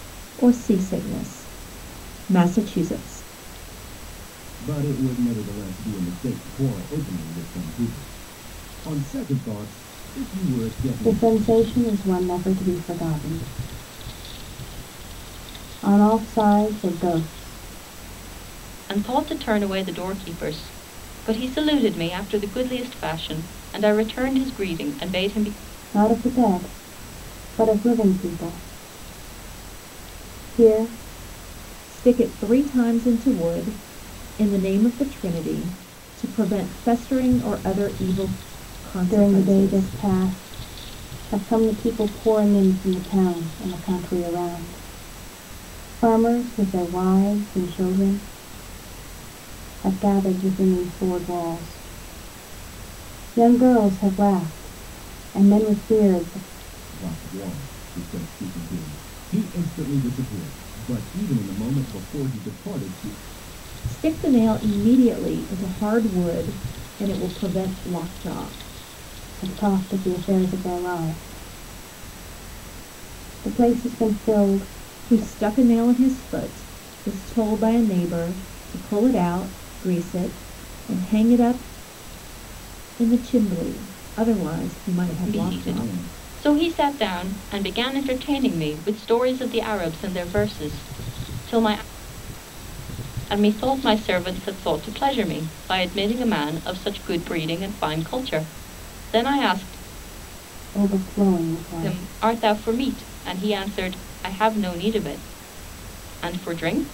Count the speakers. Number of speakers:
four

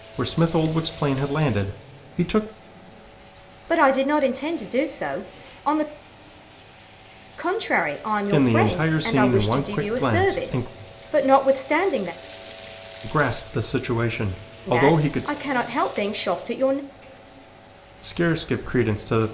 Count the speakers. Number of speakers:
two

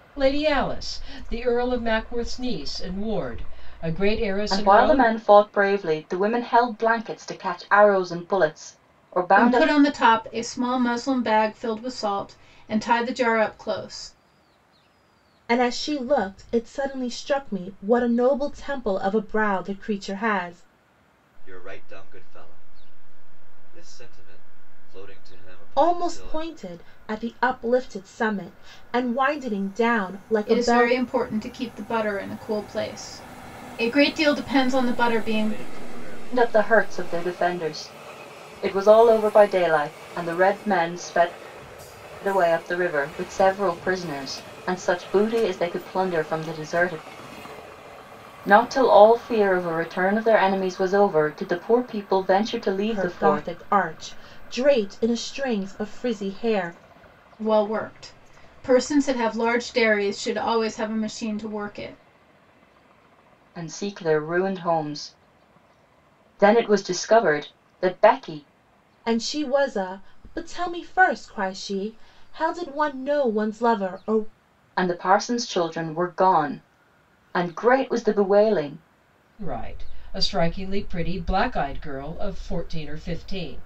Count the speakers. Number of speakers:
five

